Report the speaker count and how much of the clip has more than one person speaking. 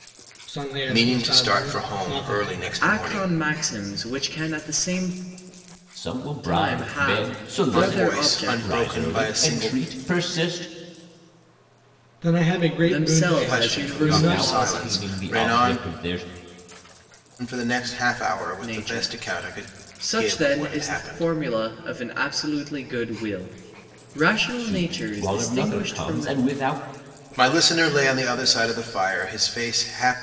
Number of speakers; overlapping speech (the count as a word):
four, about 42%